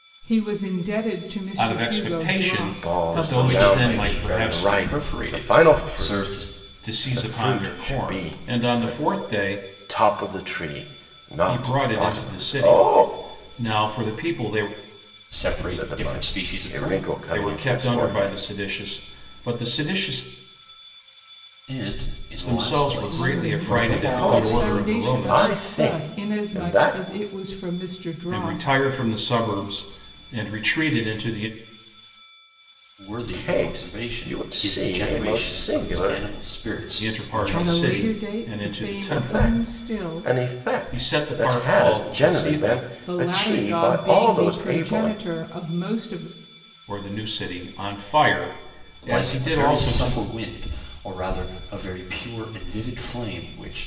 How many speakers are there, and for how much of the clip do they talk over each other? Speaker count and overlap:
4, about 52%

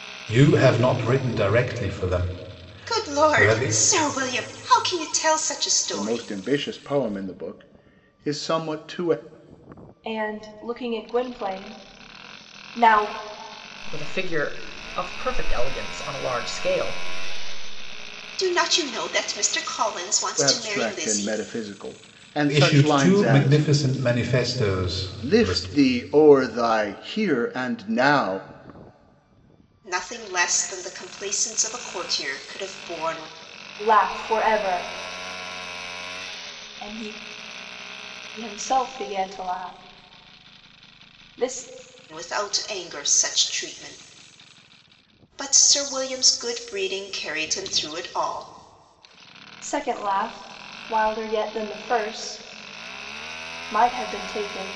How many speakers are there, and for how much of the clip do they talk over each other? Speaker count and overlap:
5, about 7%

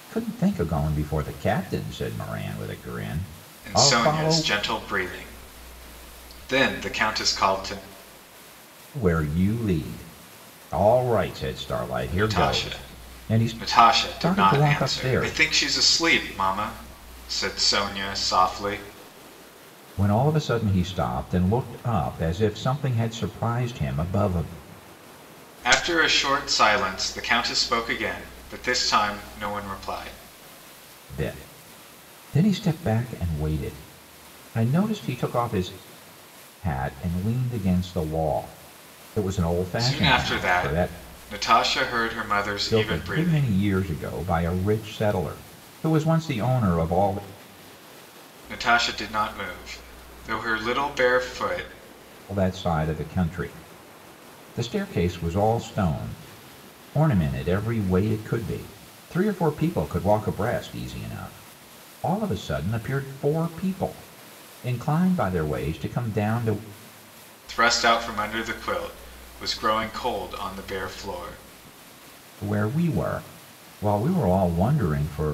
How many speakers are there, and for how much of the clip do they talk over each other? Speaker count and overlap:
2, about 8%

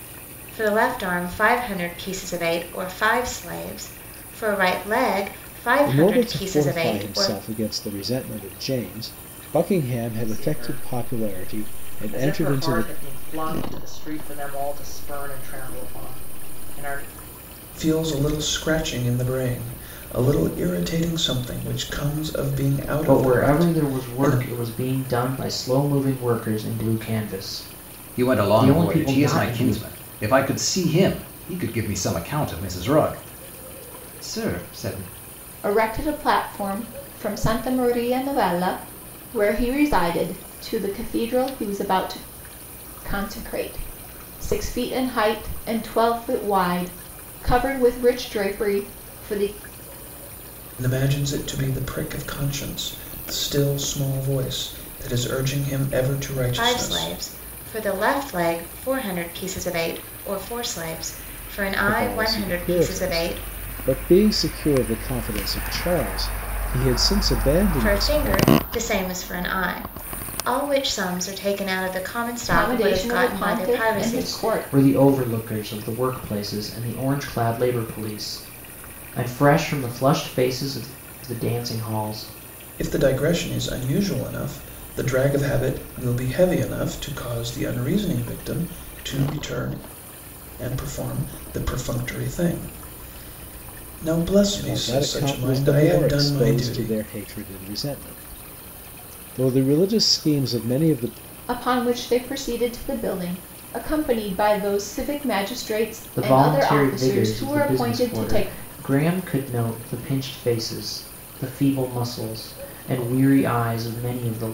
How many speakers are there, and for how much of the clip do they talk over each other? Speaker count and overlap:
7, about 16%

